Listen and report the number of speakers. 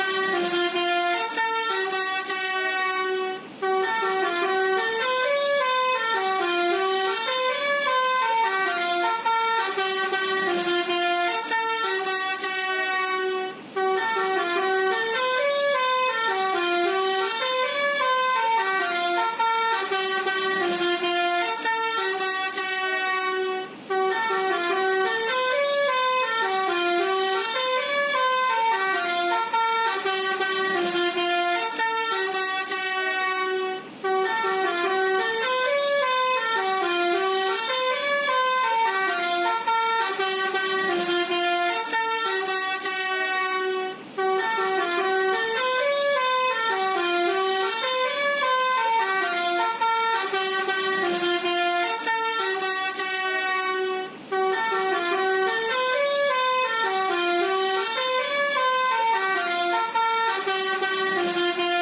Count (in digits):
0